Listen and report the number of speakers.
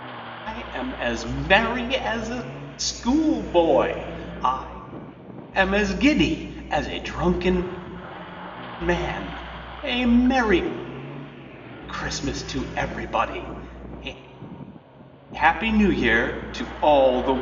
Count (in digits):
1